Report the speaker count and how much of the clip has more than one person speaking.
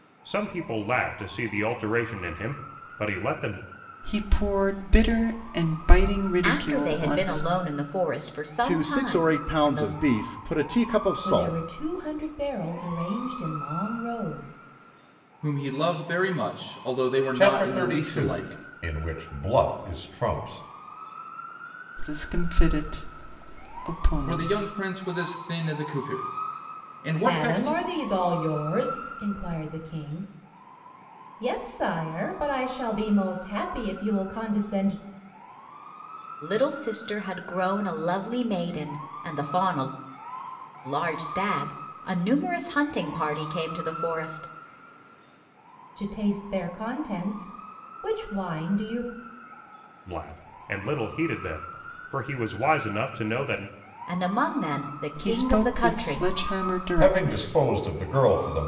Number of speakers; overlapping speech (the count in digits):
7, about 12%